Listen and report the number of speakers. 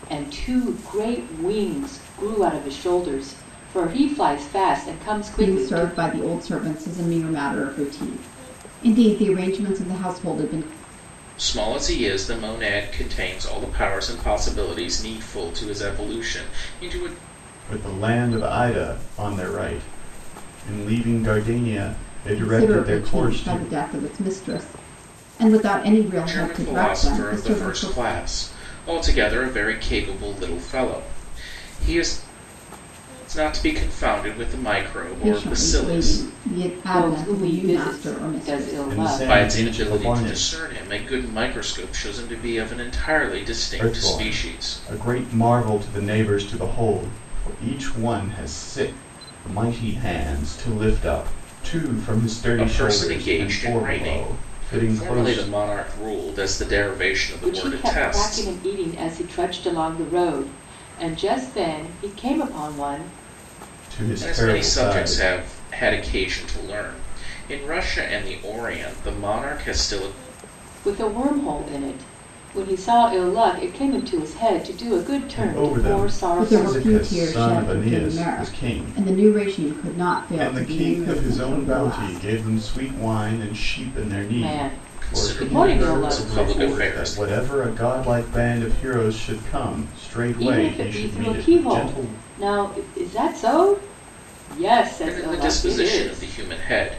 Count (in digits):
4